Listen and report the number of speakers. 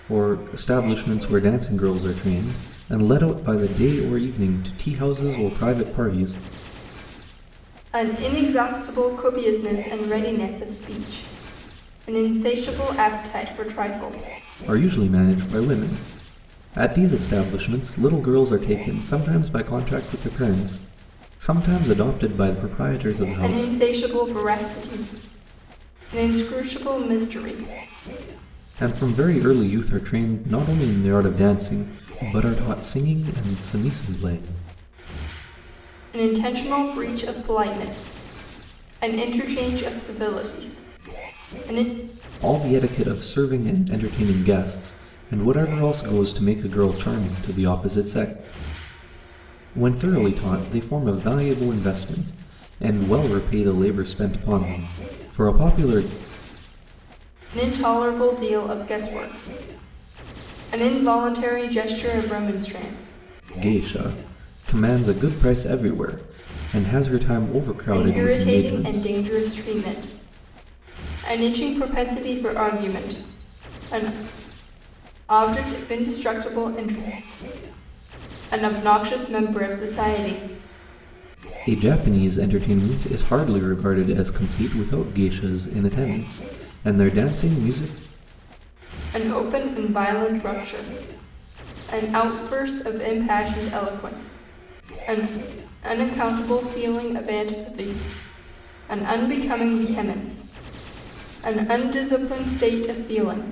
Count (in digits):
2